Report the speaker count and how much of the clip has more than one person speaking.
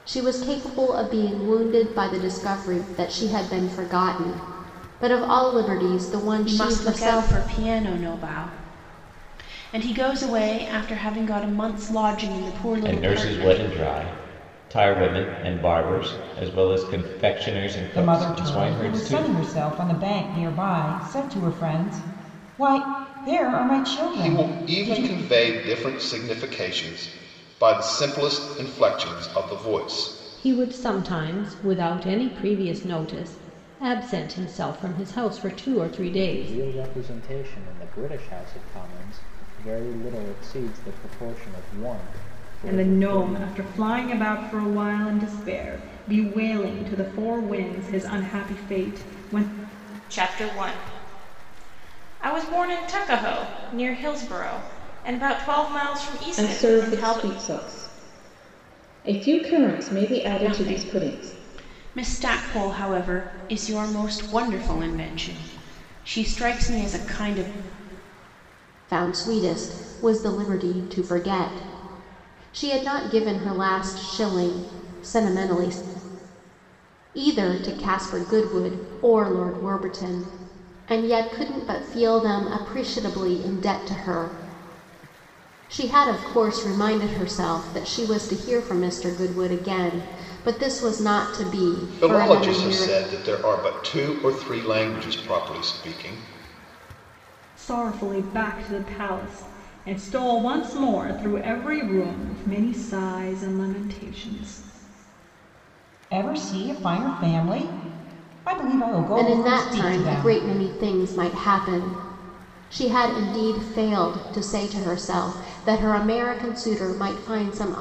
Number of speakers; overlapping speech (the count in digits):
10, about 9%